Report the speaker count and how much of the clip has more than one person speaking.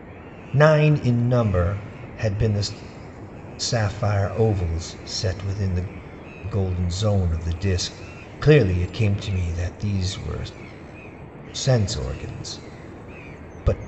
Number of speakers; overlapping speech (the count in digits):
1, no overlap